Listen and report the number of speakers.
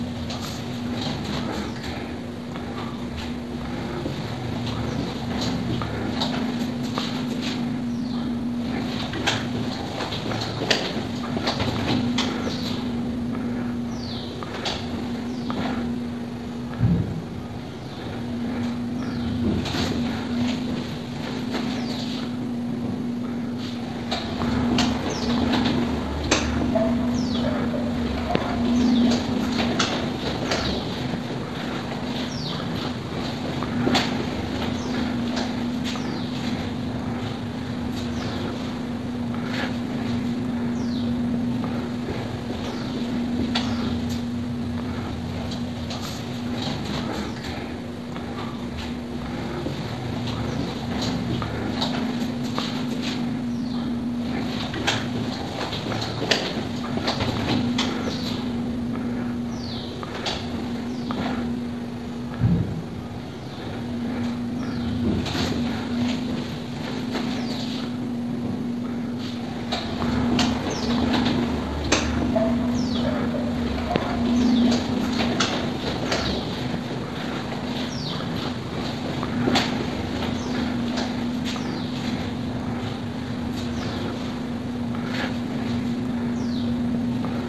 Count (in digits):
0